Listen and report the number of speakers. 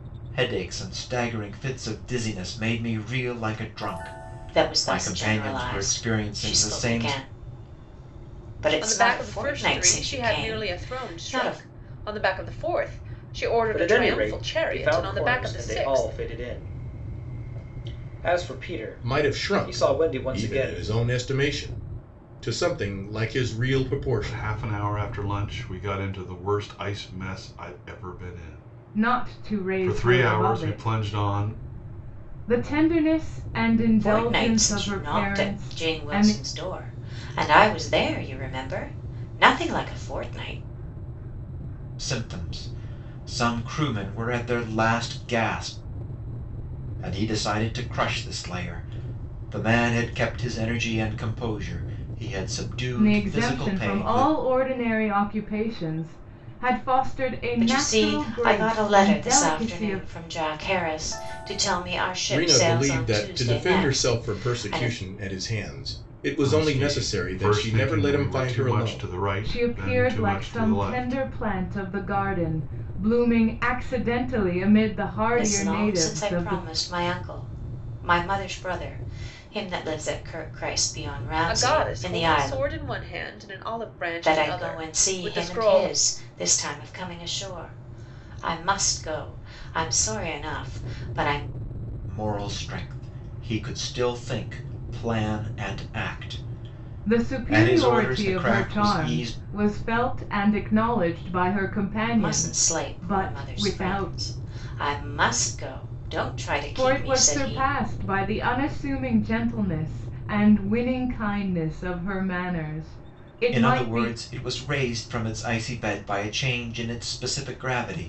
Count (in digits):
7